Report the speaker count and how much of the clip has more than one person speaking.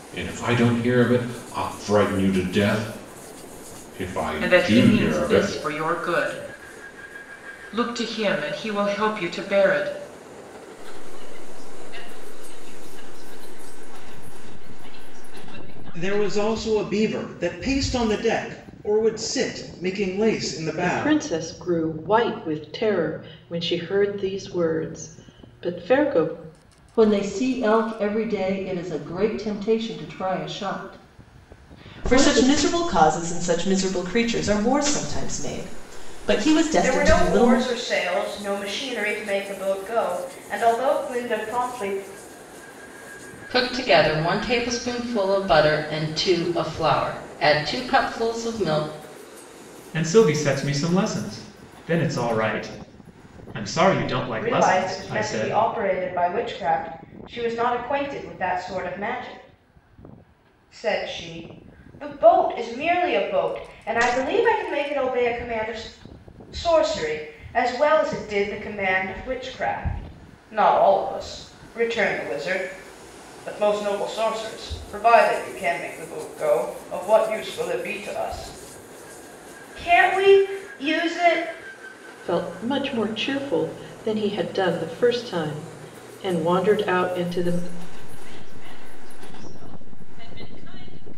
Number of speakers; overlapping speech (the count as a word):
ten, about 6%